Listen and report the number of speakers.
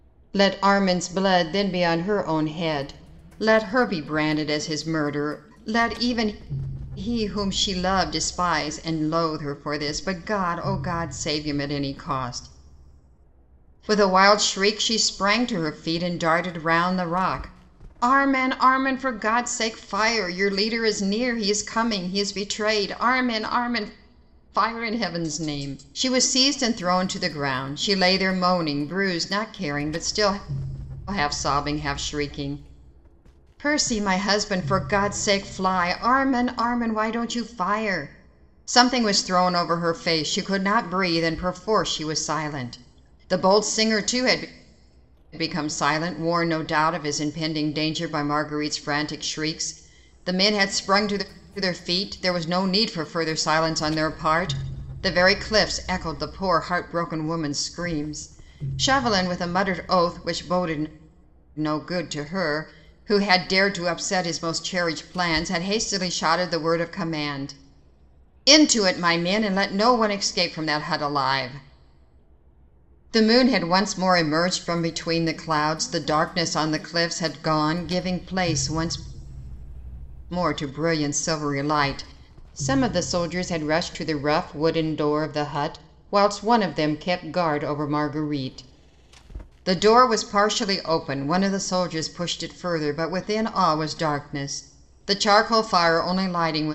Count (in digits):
1